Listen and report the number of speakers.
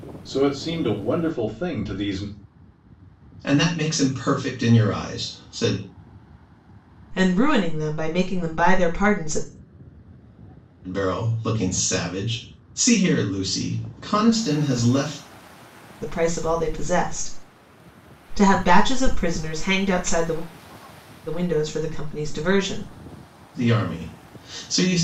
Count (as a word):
three